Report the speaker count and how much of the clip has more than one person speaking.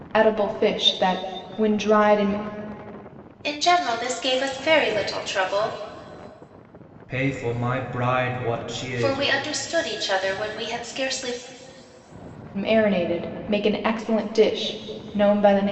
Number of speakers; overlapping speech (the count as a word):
three, about 2%